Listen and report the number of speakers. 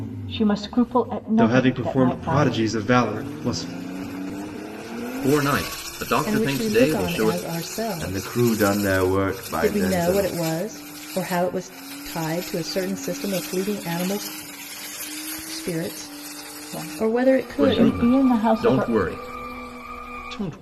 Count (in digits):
5